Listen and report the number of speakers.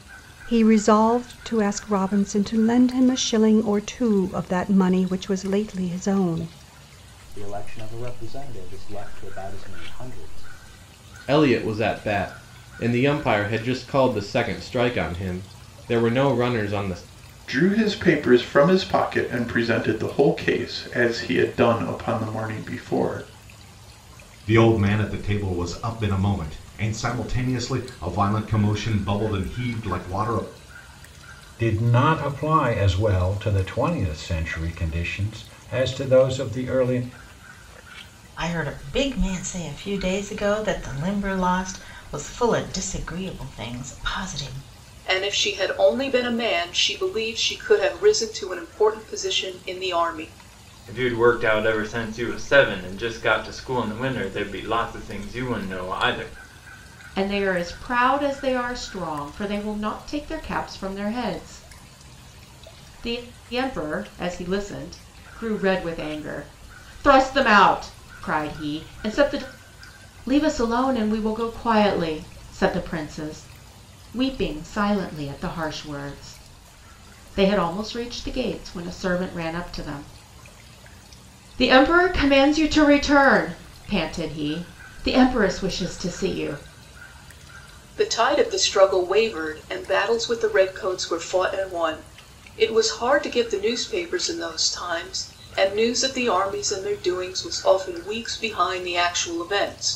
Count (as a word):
ten